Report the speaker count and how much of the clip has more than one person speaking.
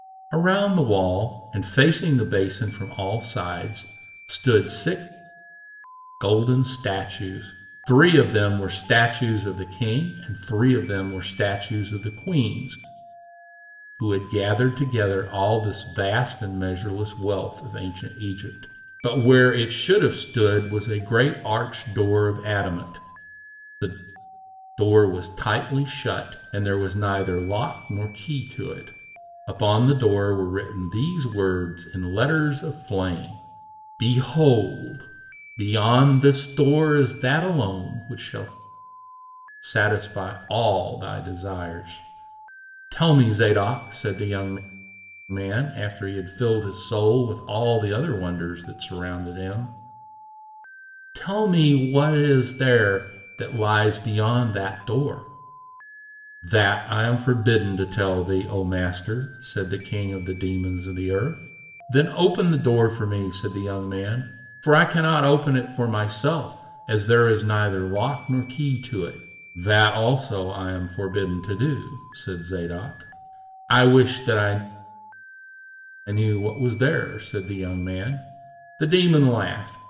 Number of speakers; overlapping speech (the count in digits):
1, no overlap